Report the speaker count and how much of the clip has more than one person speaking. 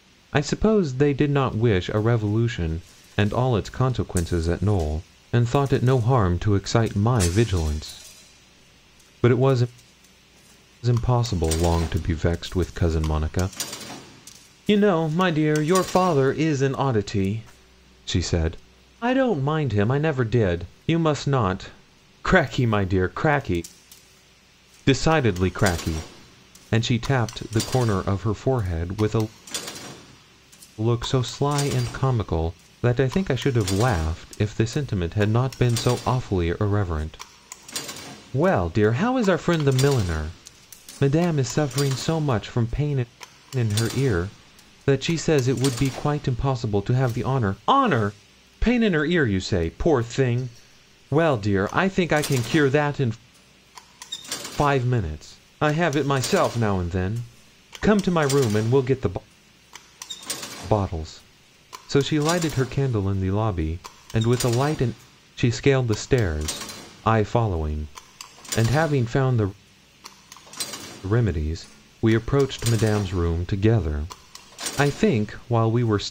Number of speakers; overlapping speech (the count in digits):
1, no overlap